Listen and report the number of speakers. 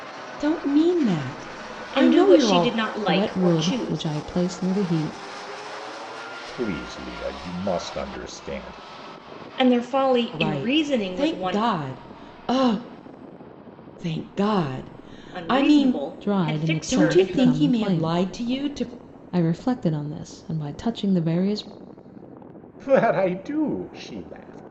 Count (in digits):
4